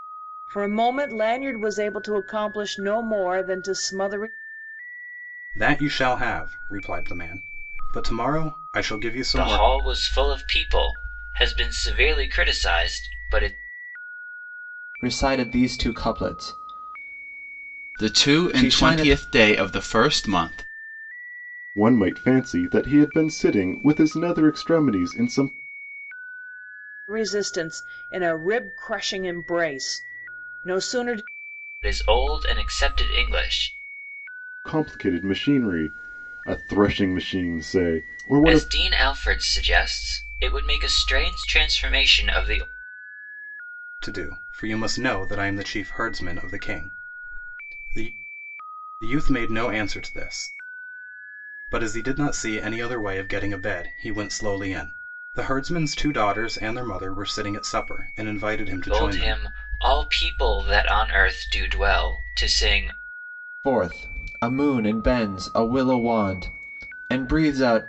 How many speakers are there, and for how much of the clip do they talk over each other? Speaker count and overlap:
six, about 4%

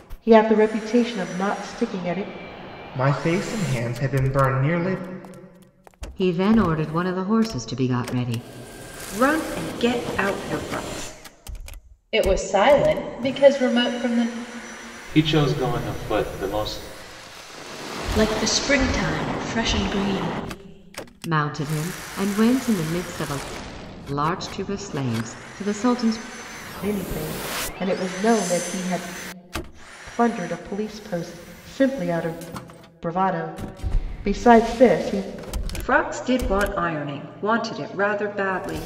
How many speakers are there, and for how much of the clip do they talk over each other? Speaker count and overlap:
seven, no overlap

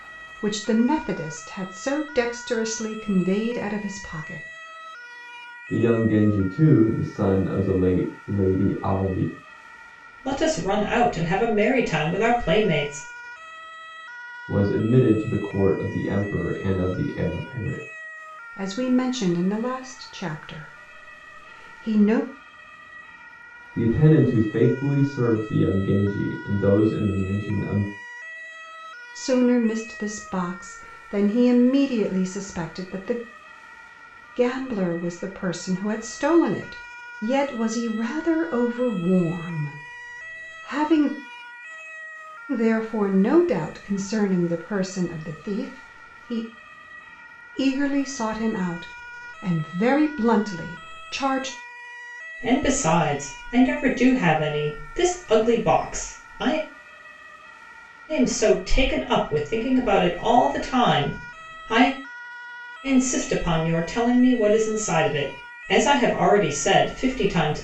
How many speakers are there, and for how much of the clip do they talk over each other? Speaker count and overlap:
three, no overlap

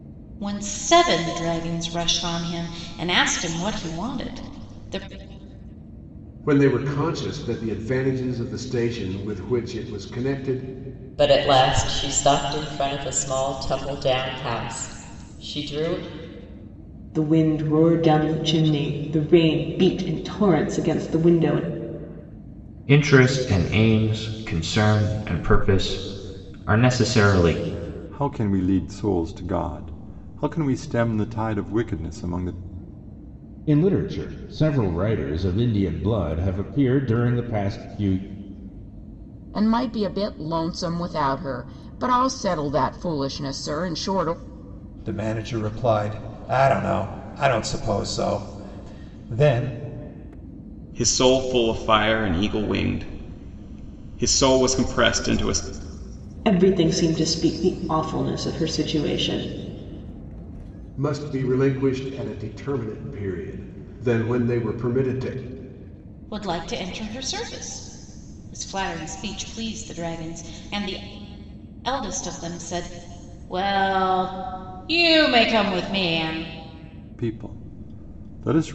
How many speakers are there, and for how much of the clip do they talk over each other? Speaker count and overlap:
ten, no overlap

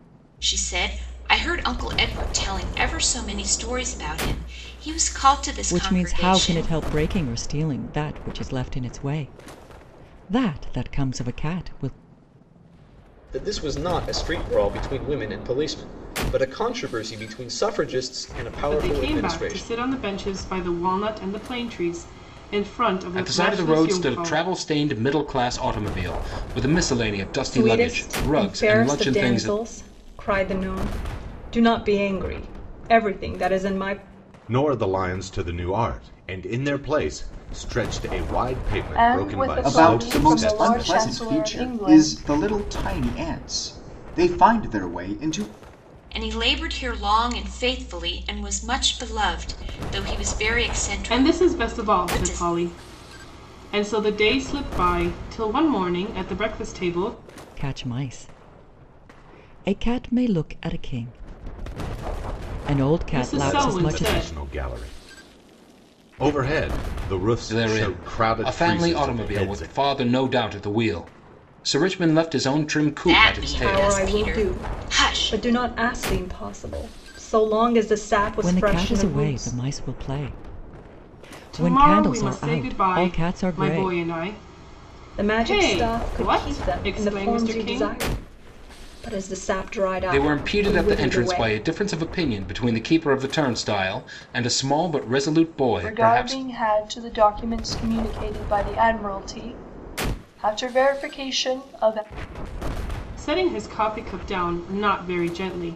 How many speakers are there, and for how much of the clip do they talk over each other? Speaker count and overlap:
nine, about 24%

